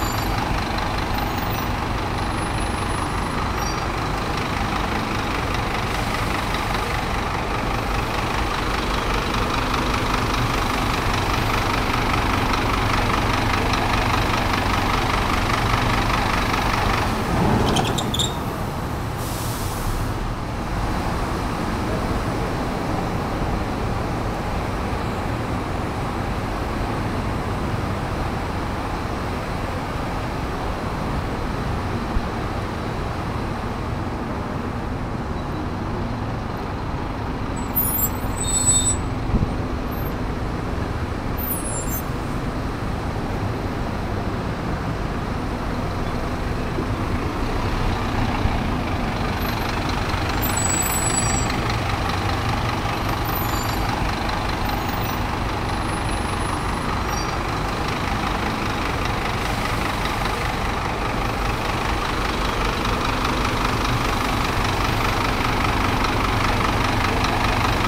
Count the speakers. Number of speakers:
zero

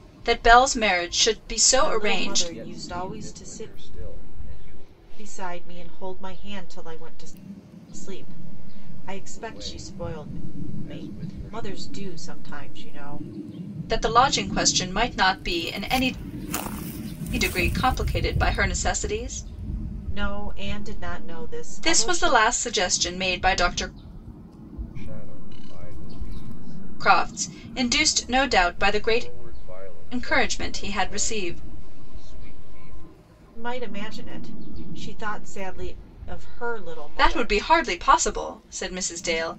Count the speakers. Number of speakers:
three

